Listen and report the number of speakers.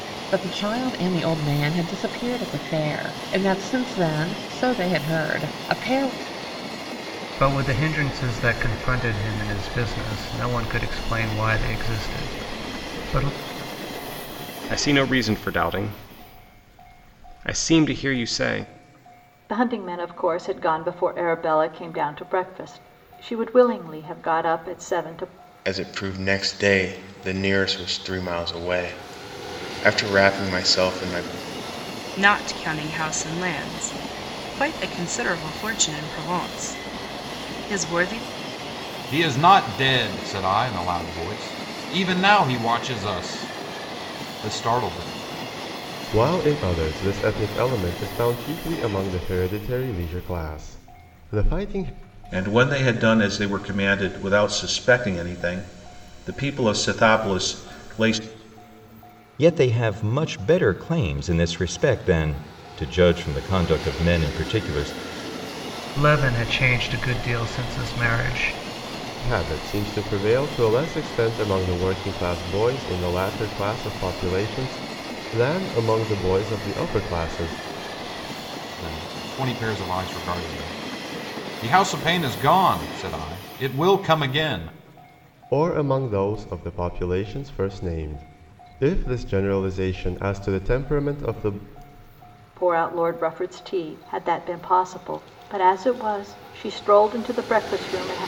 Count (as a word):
ten